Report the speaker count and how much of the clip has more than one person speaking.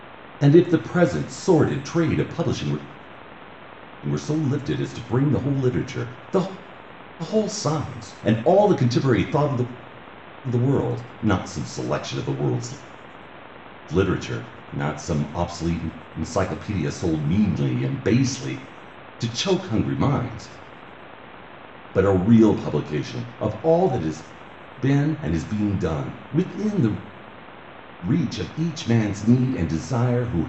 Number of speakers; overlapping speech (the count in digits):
1, no overlap